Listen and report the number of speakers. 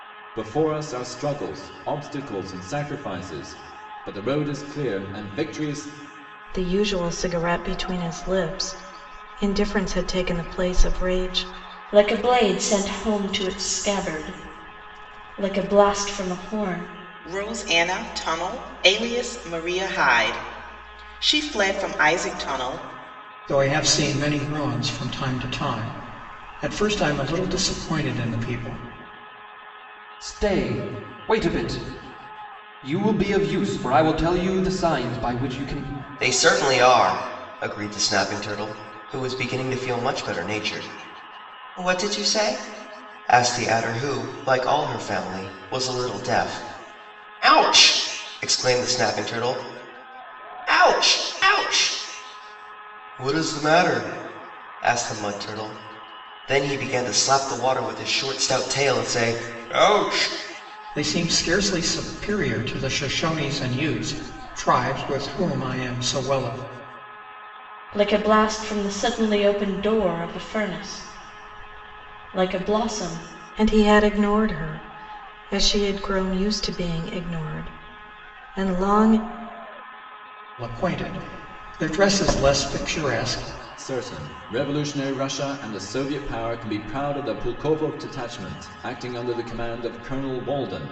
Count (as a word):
seven